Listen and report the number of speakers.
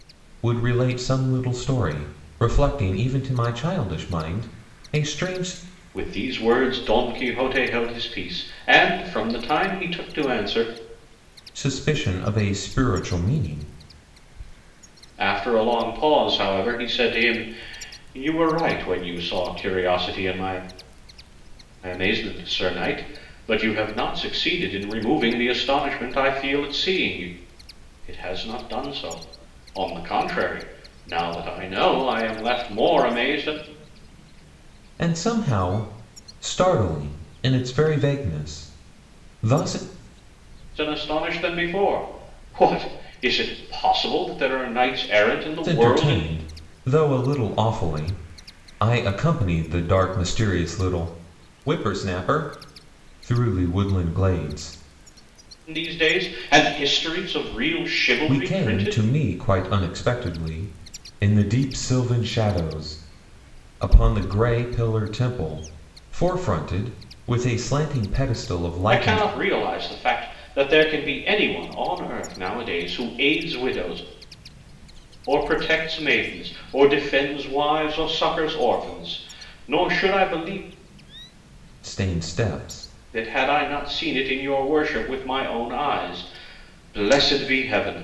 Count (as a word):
two